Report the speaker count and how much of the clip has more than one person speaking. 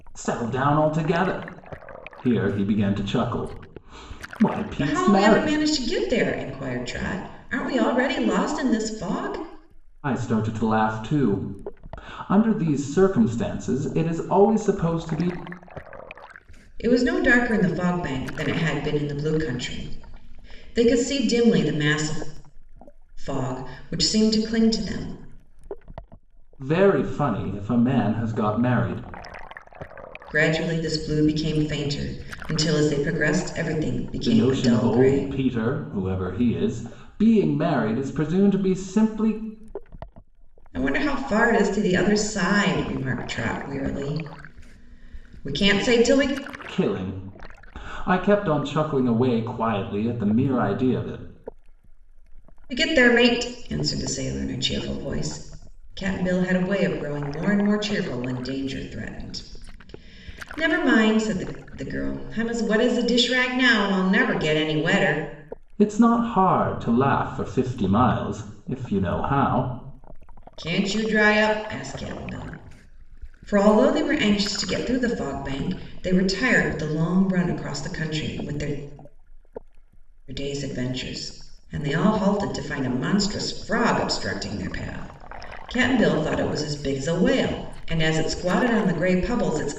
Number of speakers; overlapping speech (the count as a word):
two, about 2%